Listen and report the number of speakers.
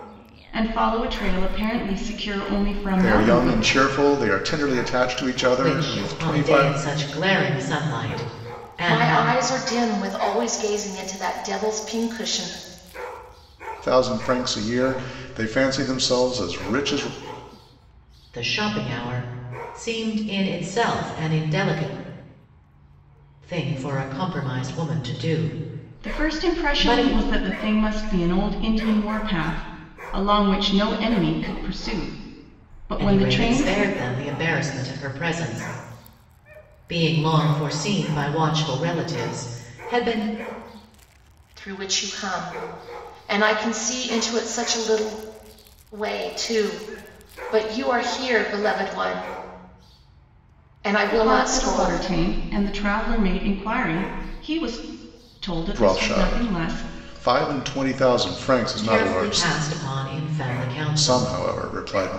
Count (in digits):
4